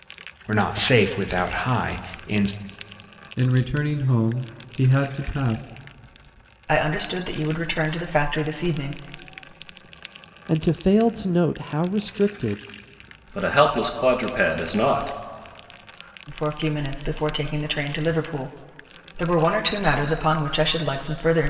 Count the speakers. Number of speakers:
5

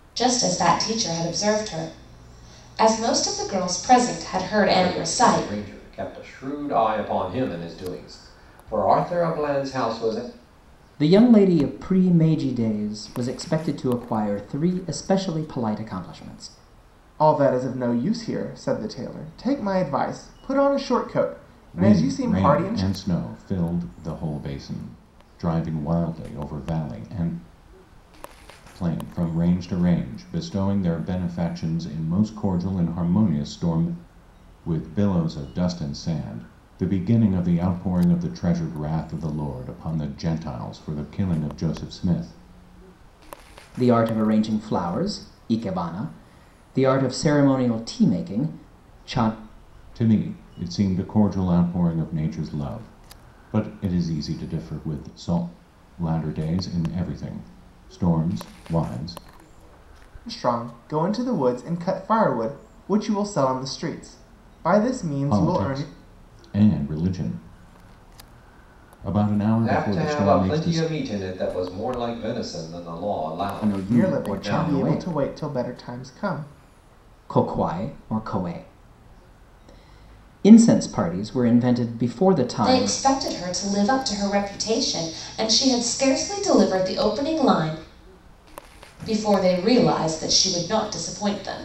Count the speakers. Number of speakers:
5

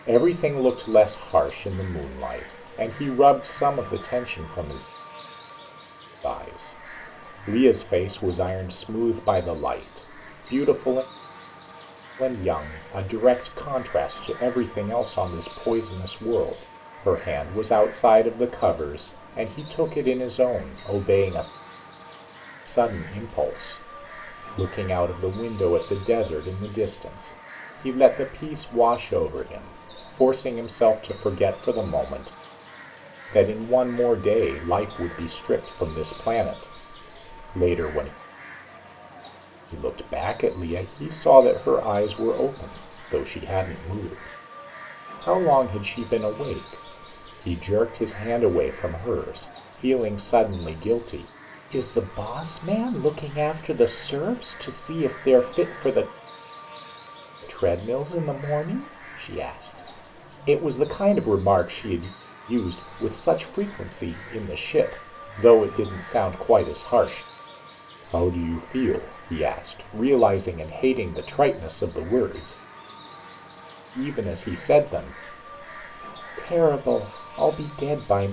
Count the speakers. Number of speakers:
1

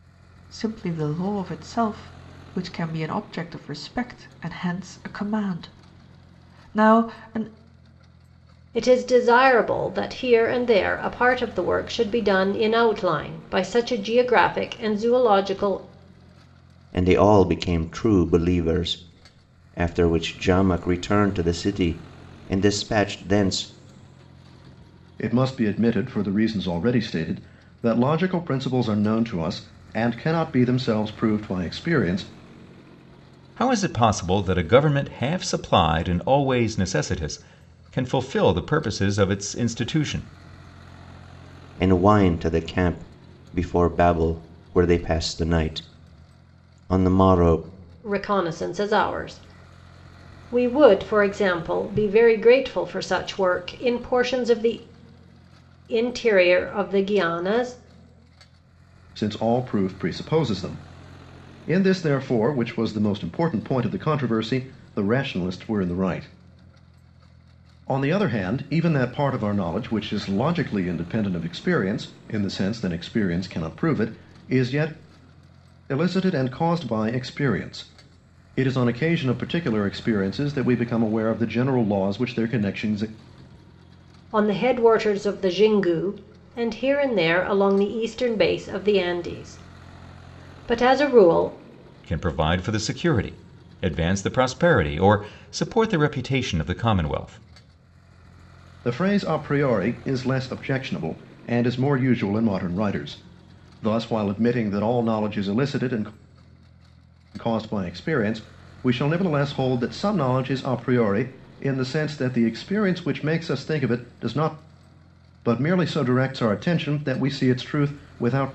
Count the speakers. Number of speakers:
5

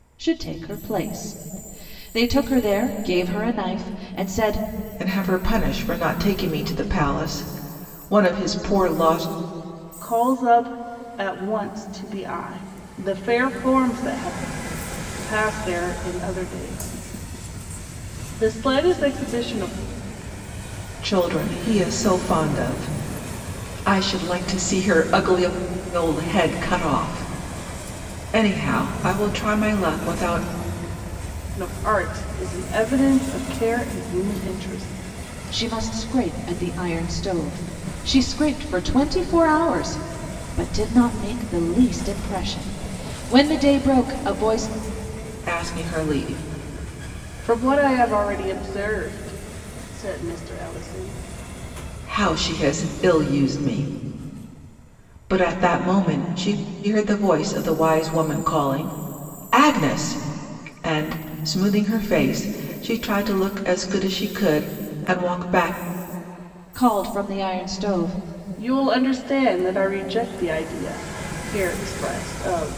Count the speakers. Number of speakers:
3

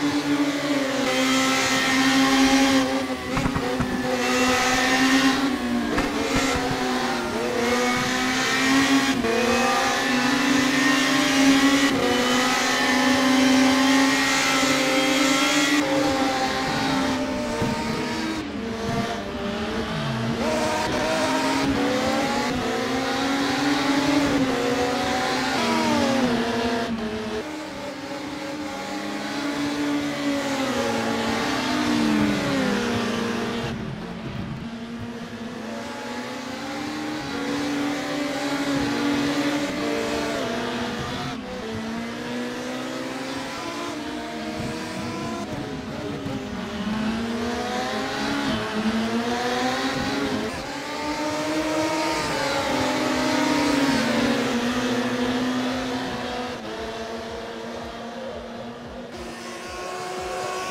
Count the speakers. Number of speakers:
0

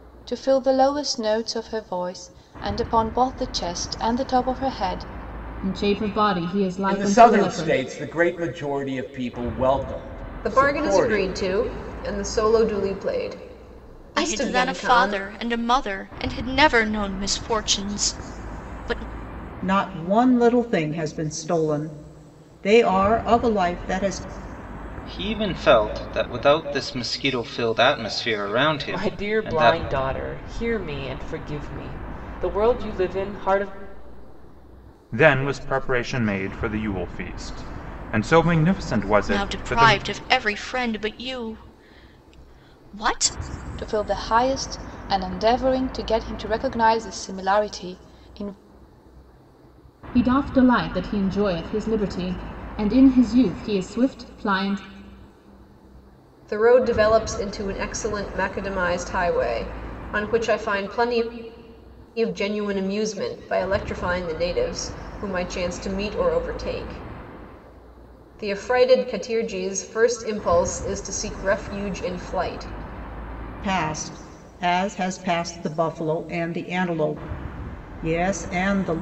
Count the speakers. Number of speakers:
9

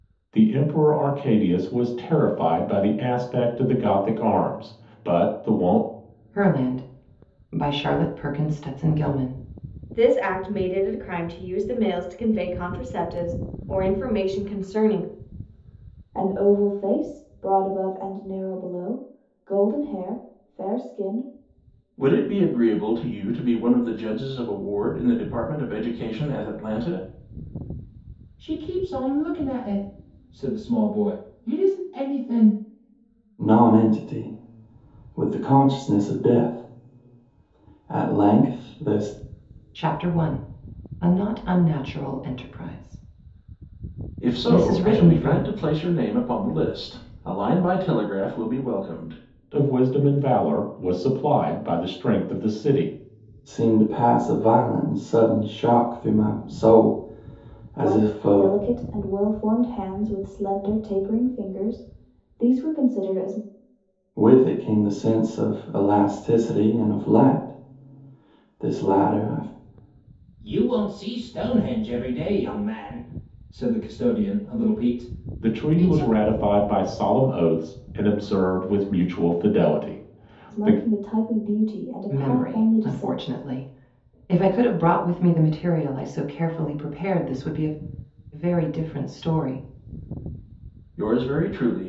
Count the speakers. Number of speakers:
7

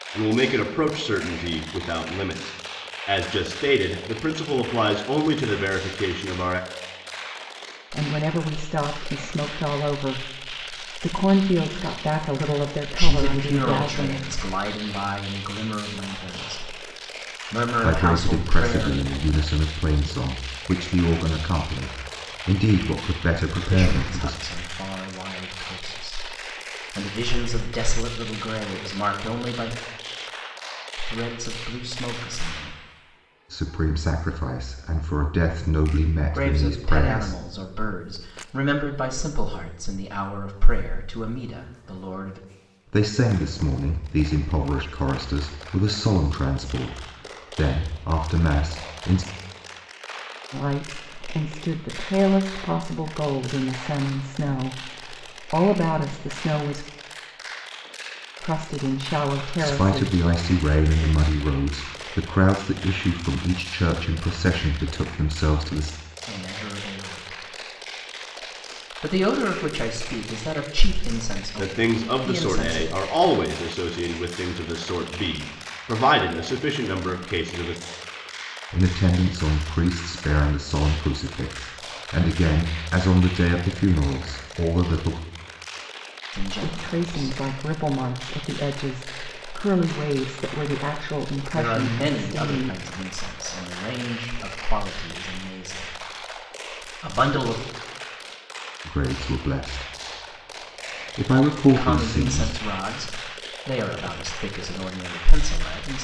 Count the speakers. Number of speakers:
4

